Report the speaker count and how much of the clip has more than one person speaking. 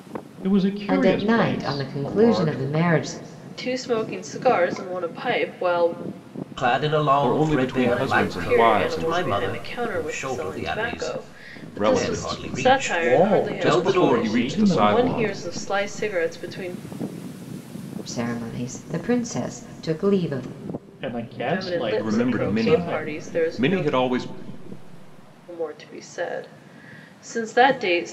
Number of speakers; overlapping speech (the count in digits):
5, about 43%